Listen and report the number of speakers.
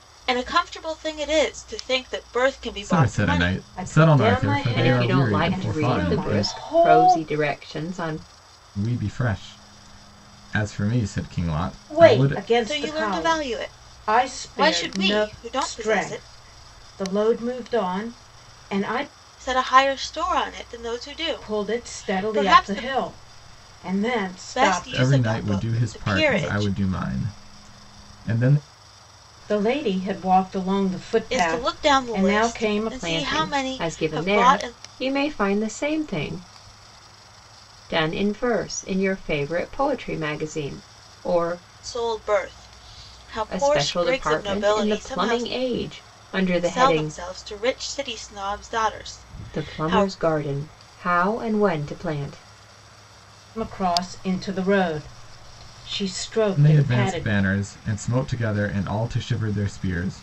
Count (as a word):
four